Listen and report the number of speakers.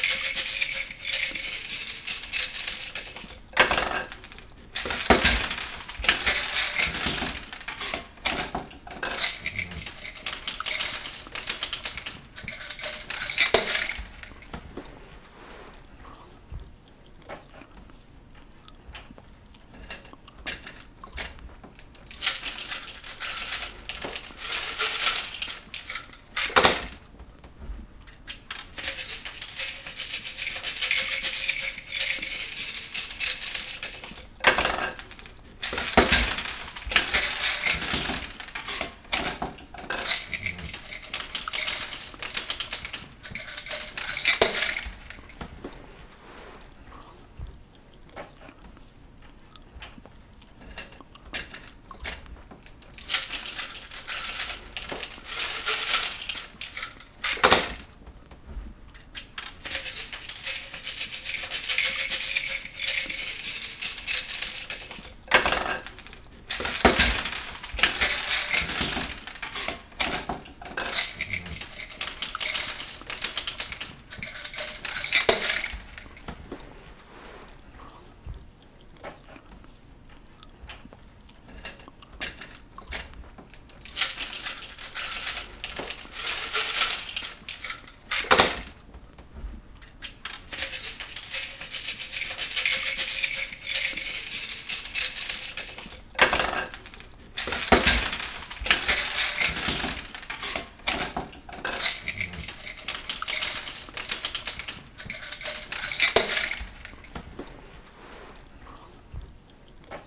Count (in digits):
0